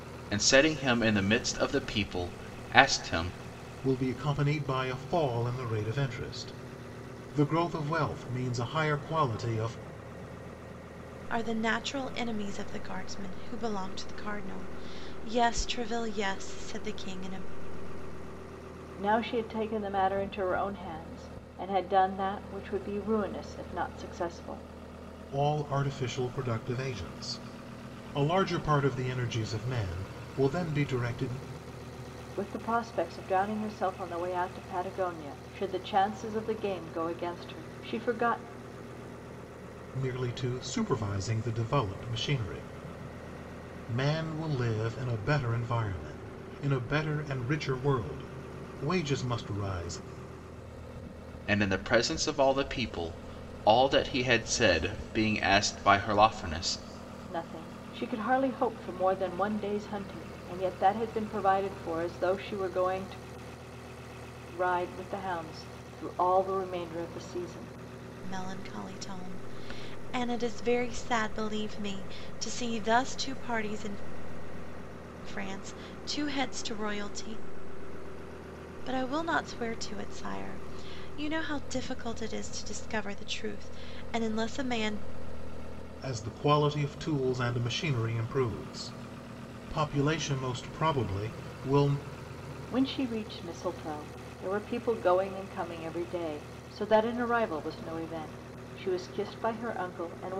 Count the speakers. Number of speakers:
four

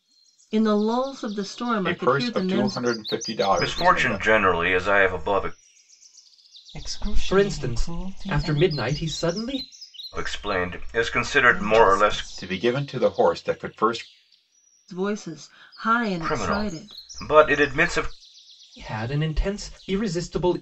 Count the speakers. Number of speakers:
five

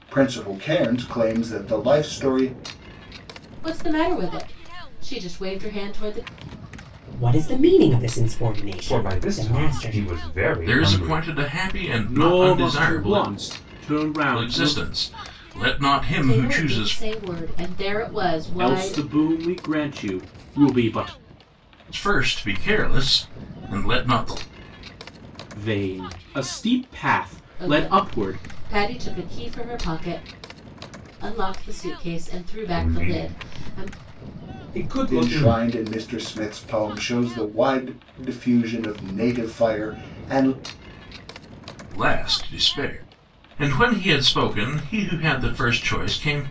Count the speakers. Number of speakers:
six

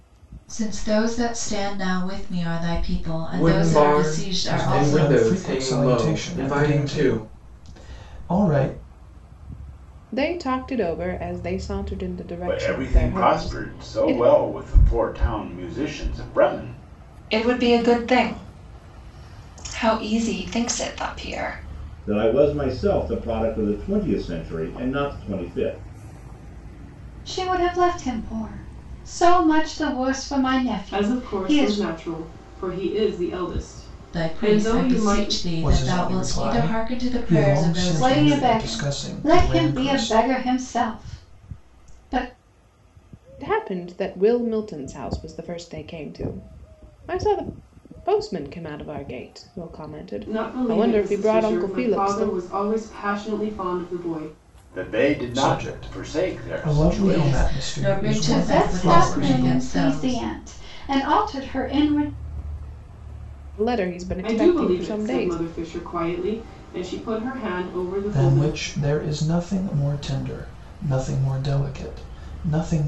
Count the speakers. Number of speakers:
nine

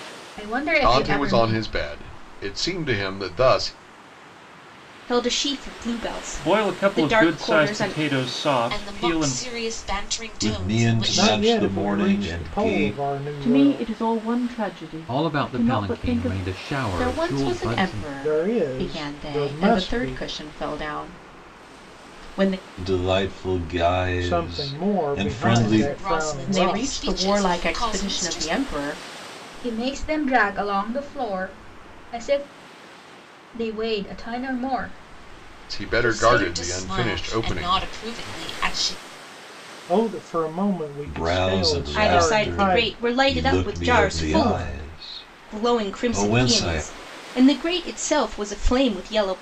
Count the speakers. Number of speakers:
ten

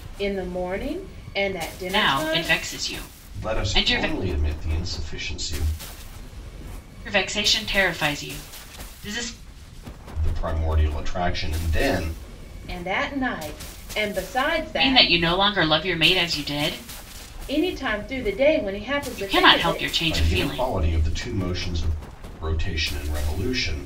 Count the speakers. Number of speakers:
three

